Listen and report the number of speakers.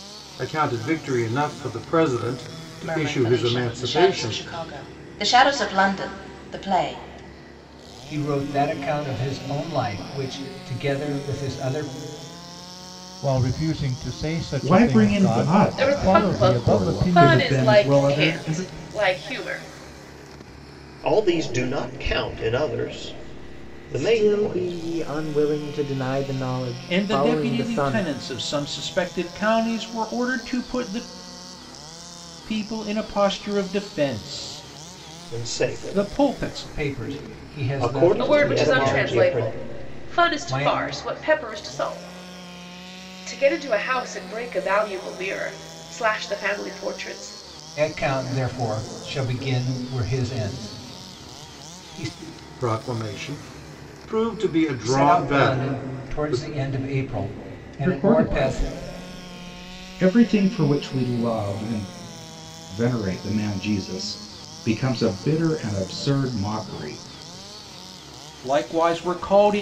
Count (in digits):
9